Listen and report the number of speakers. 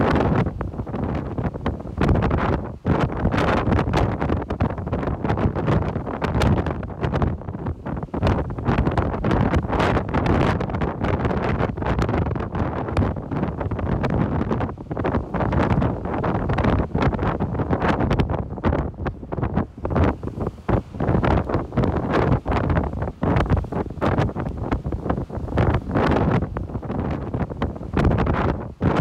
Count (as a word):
zero